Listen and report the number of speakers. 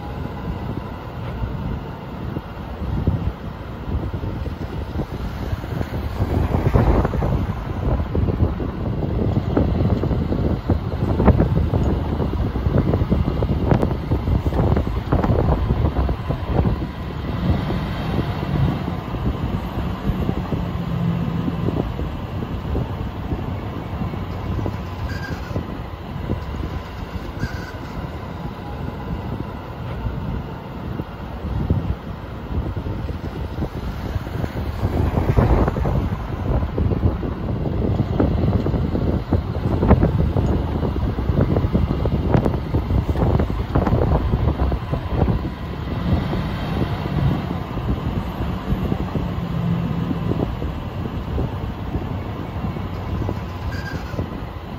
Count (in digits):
0